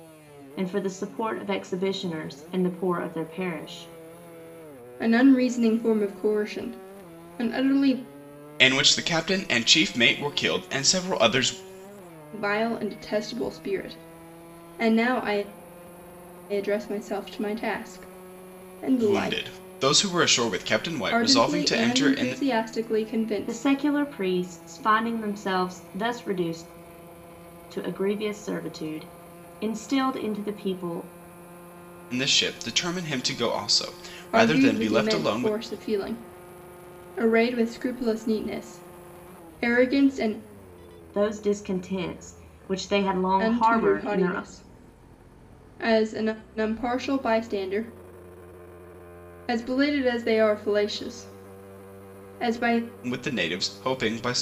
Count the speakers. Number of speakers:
3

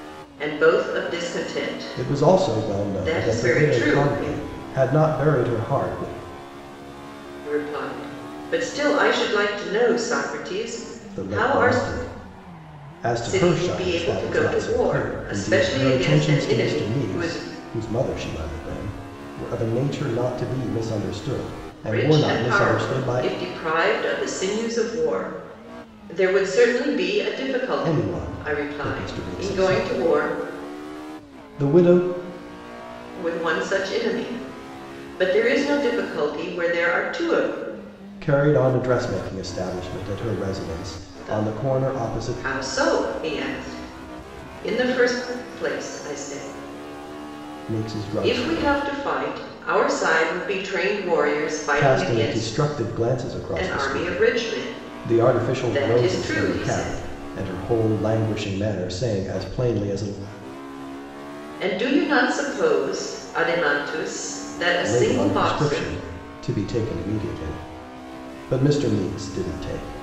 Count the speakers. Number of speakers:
2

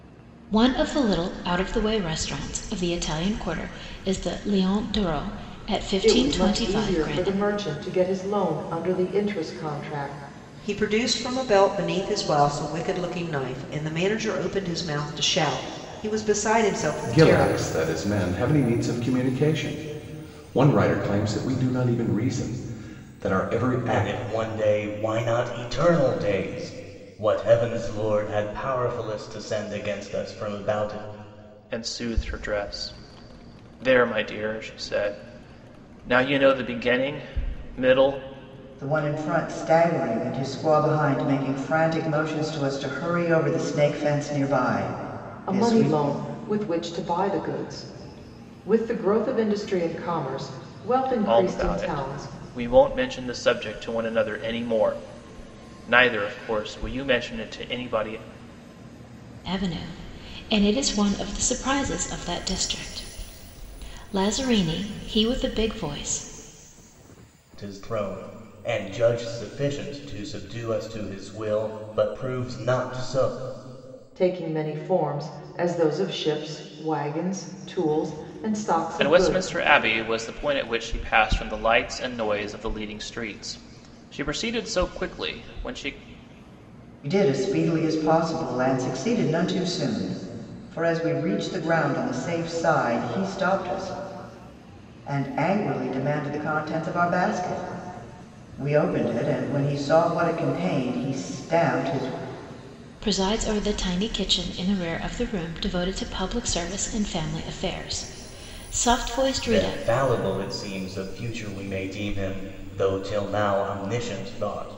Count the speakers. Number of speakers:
7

